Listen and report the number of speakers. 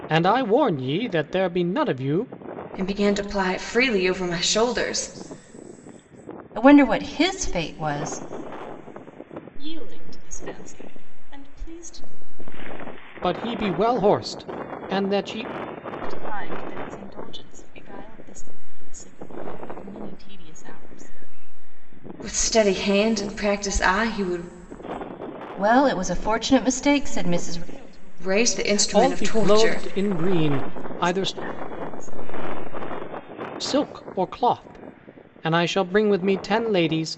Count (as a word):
four